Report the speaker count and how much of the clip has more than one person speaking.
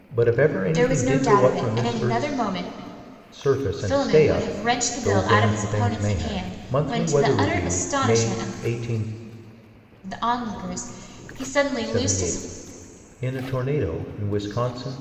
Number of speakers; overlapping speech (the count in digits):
2, about 46%